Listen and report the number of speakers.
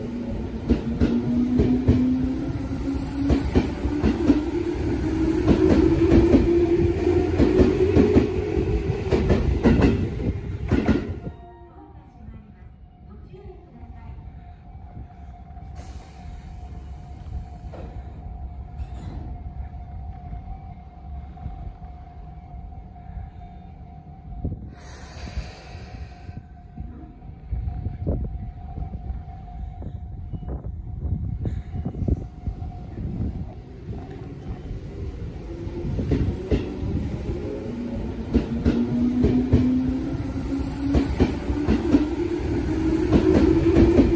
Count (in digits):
0